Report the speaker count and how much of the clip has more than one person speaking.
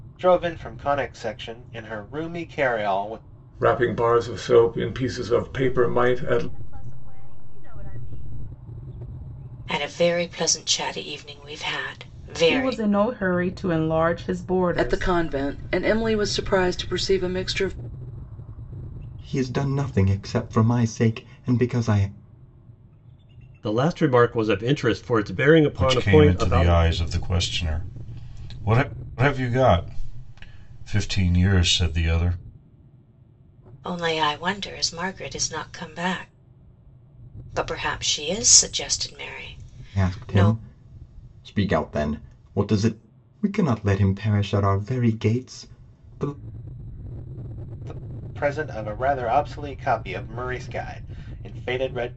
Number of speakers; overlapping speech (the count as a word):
nine, about 6%